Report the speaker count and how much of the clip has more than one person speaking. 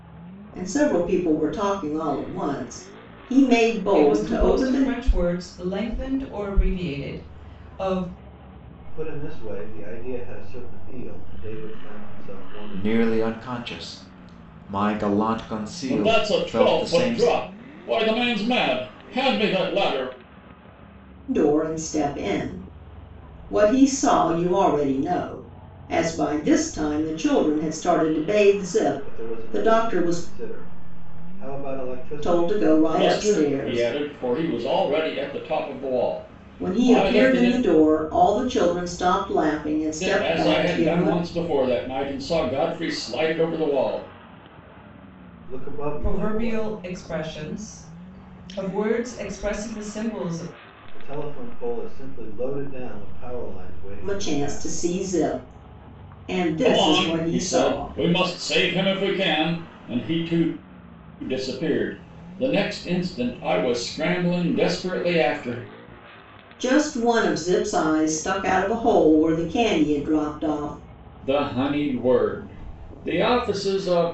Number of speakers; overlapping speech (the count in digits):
5, about 15%